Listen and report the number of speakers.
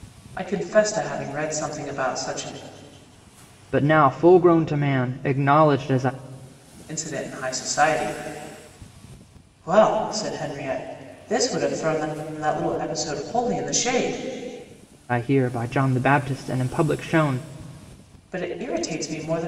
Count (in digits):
2